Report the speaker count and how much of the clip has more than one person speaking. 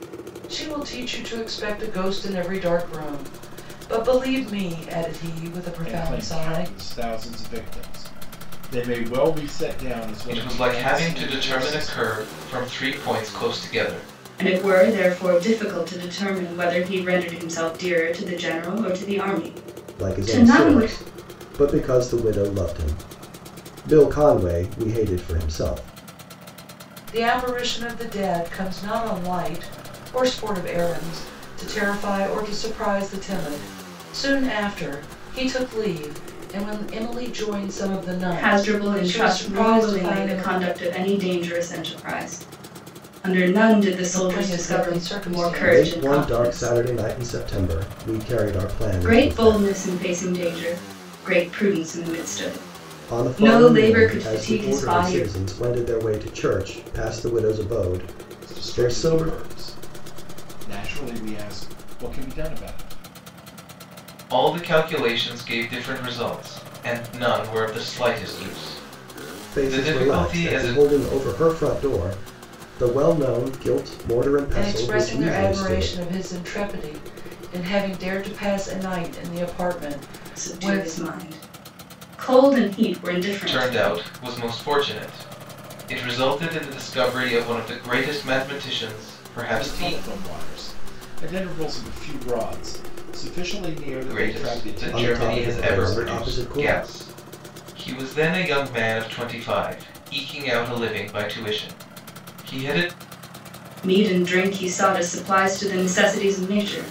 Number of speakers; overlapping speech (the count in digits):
5, about 19%